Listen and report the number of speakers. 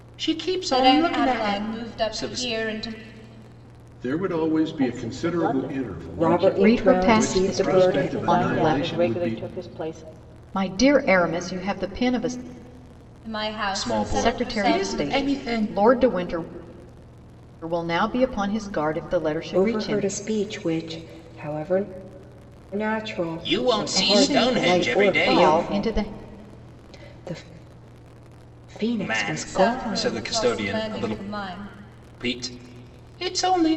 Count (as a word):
six